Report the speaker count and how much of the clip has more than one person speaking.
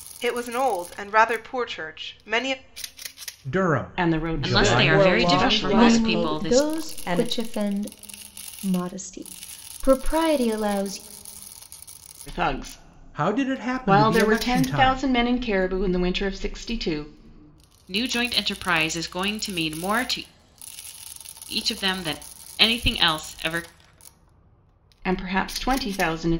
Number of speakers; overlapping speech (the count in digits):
6, about 20%